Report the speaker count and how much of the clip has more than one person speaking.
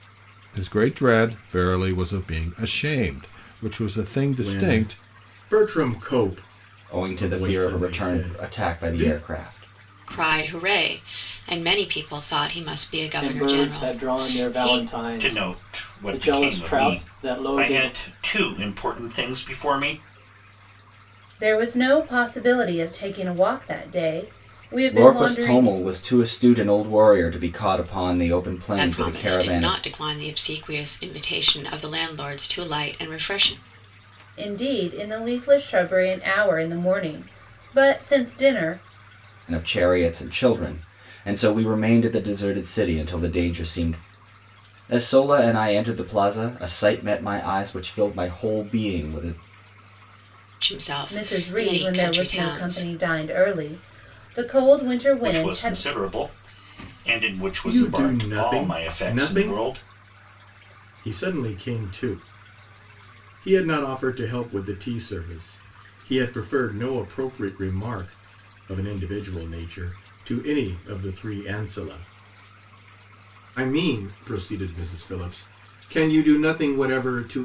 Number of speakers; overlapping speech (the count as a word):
seven, about 18%